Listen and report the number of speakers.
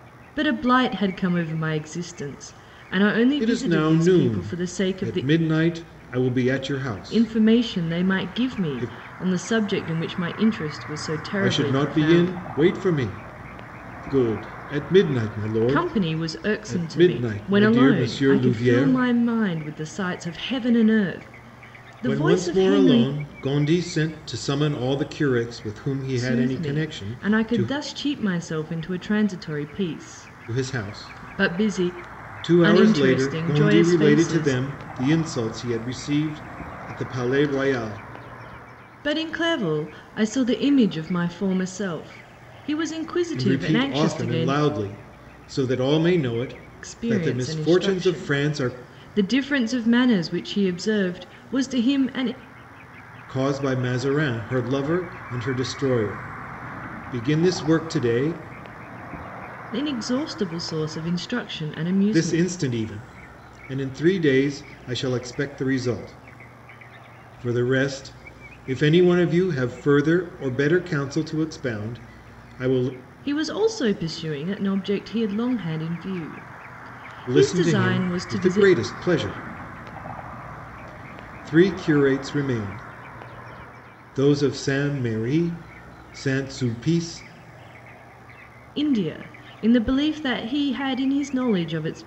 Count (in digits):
2